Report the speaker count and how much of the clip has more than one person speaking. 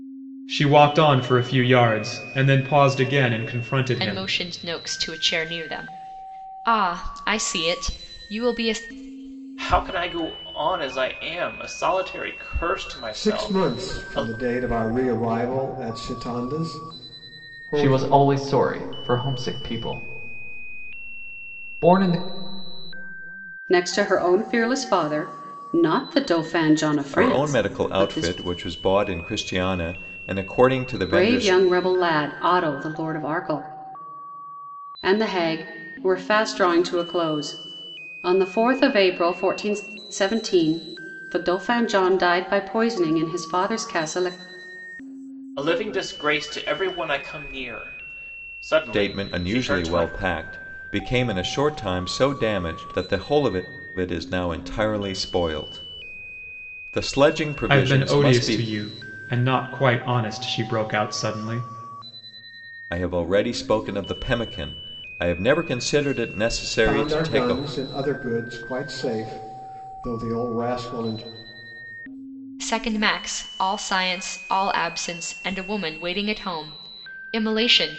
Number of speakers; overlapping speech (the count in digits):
7, about 9%